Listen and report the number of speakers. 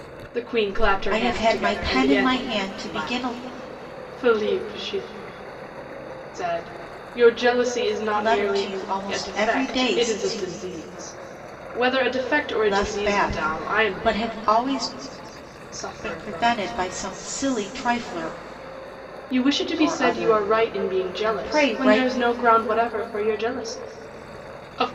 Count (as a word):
two